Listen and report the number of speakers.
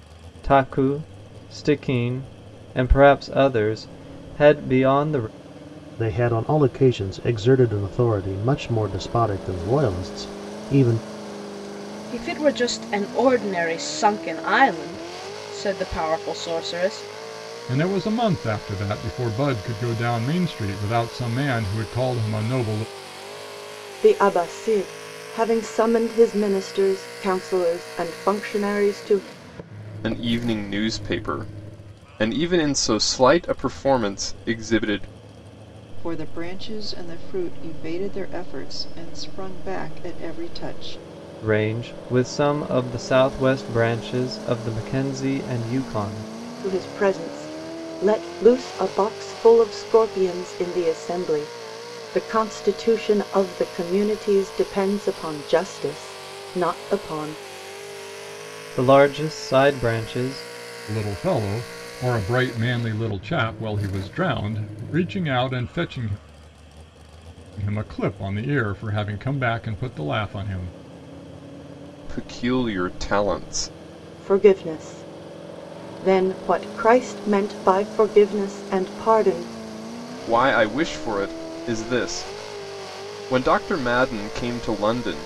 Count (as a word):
seven